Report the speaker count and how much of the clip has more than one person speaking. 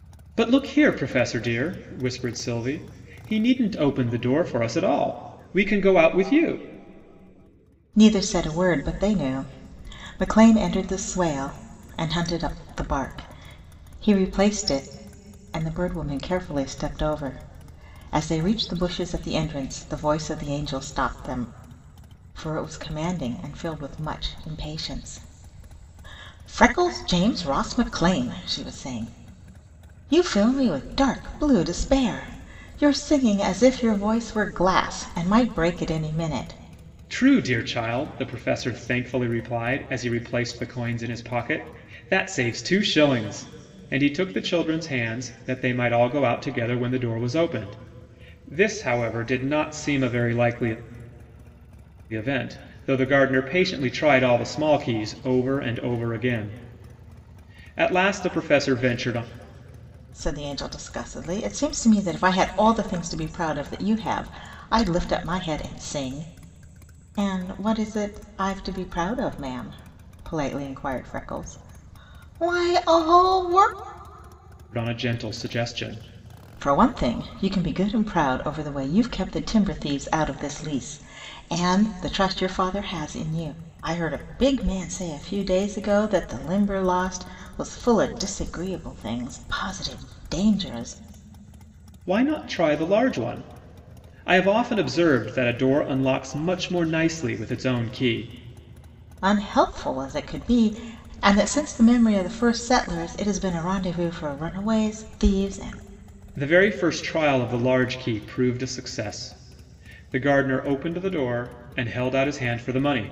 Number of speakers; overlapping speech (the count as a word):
two, no overlap